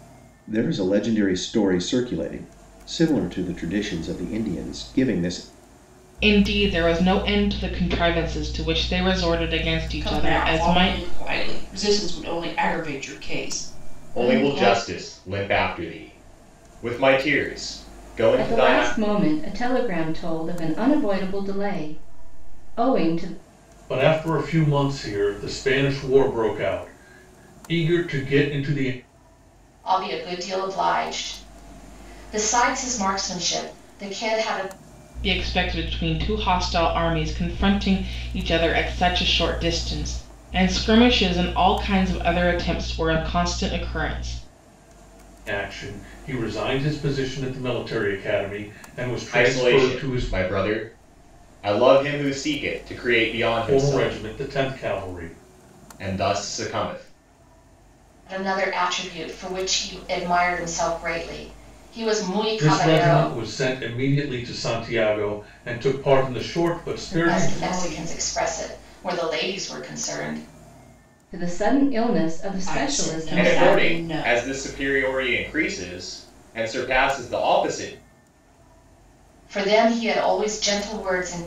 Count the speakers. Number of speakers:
7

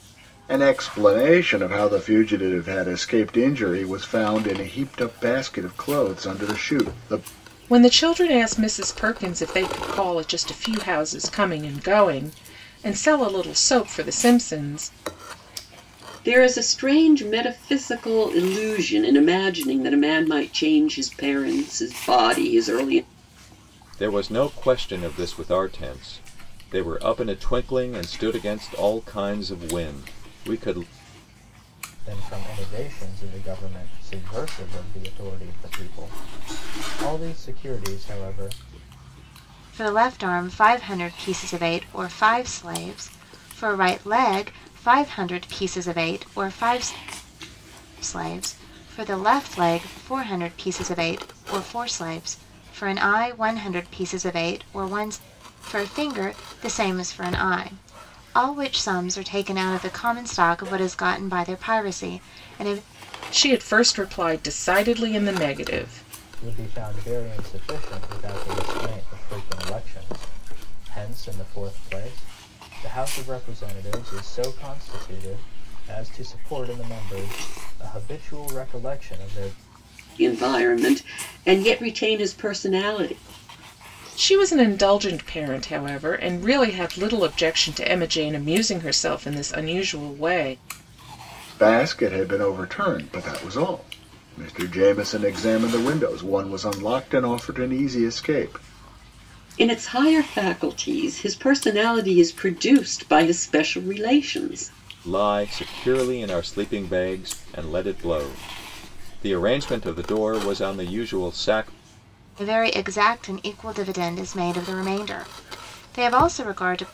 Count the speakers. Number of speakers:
6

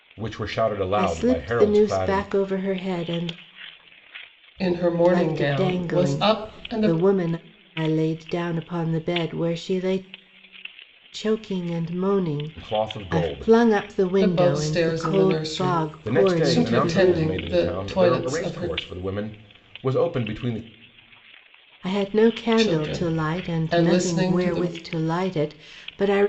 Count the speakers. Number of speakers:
3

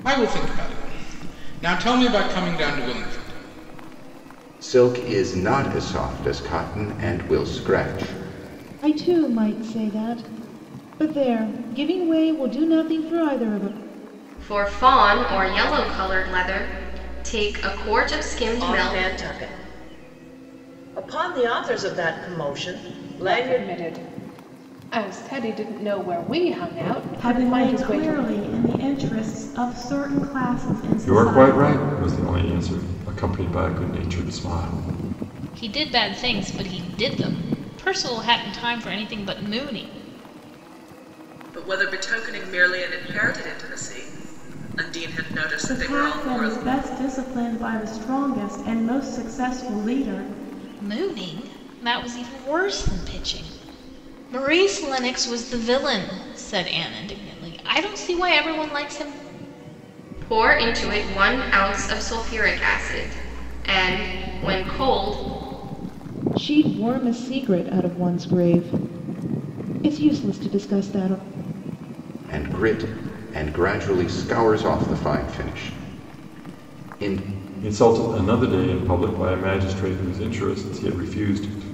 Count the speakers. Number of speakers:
10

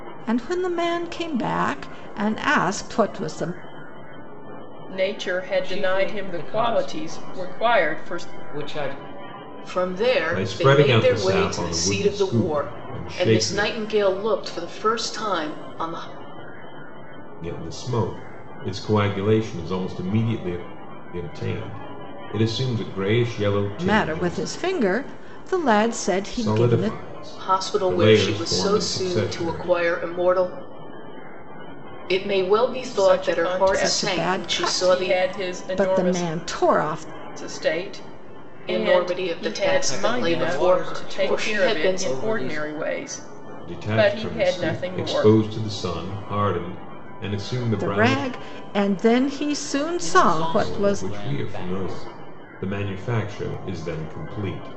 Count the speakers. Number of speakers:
5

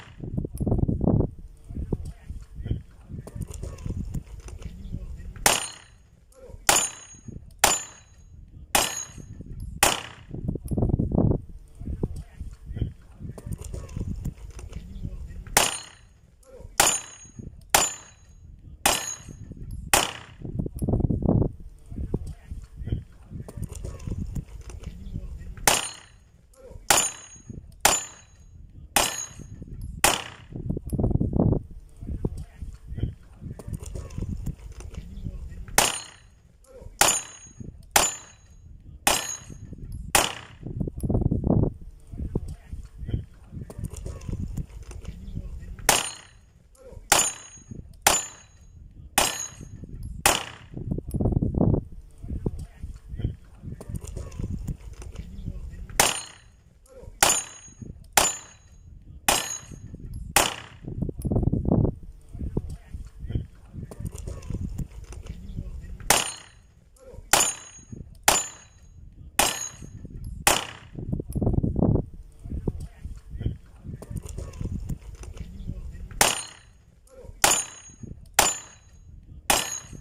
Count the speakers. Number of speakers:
0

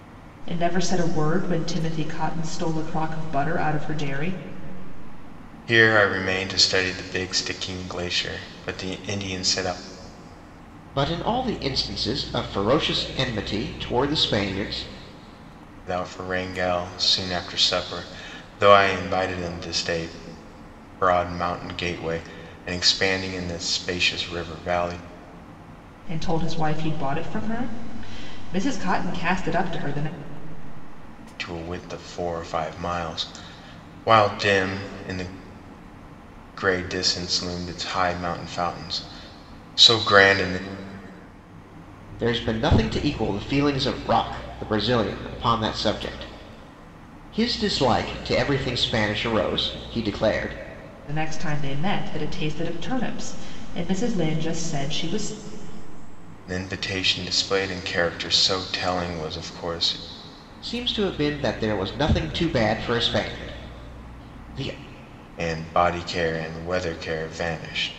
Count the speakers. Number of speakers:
3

